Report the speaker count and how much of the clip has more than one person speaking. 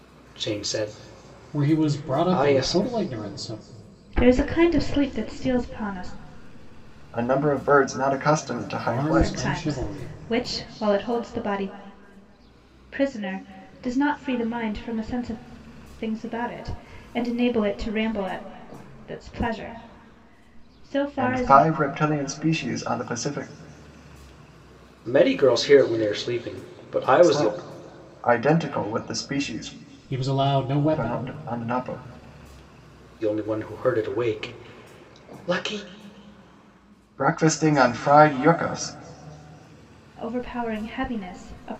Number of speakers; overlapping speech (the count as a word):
four, about 9%